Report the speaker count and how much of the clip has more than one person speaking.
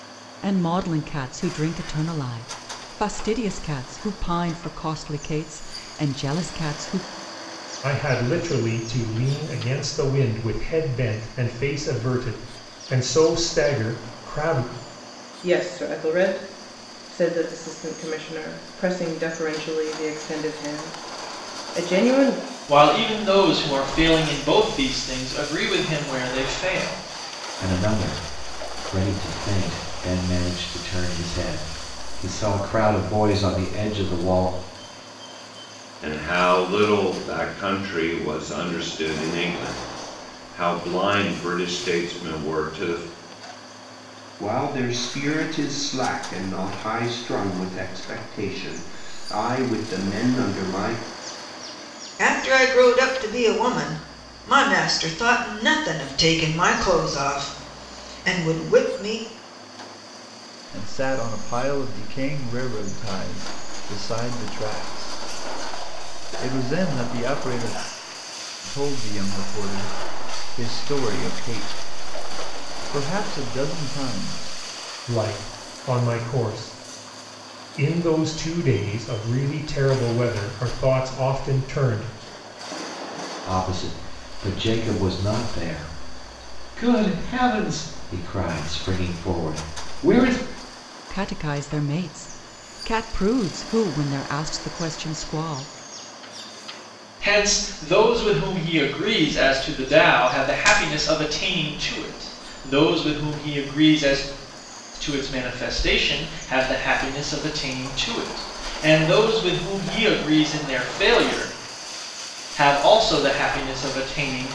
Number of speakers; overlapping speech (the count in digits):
9, no overlap